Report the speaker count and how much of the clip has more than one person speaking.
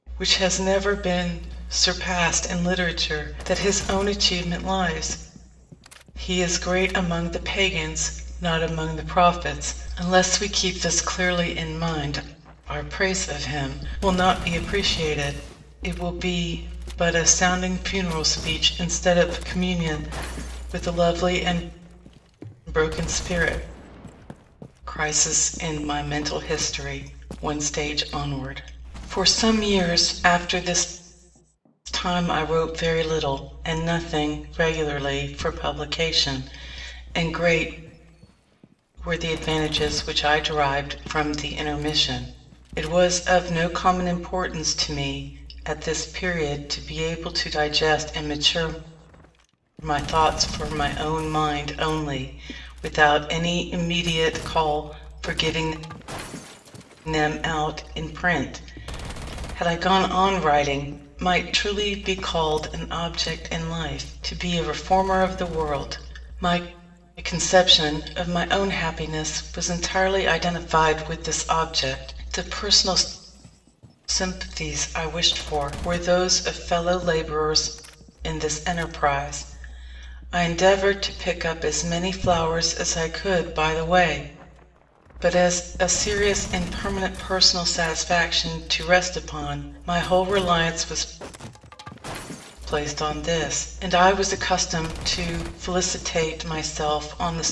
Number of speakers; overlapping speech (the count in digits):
1, no overlap